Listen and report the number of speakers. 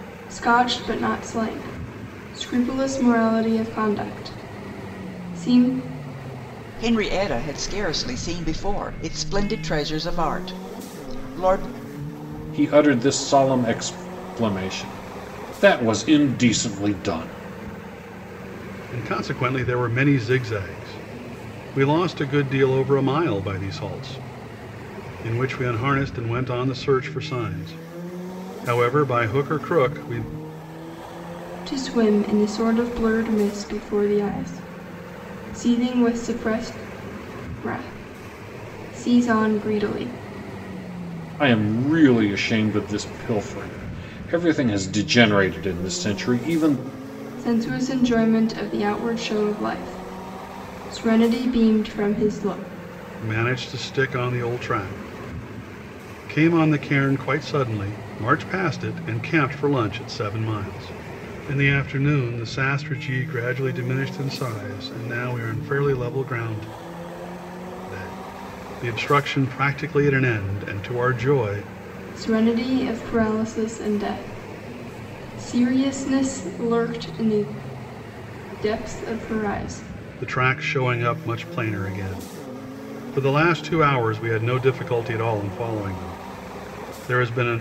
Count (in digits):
4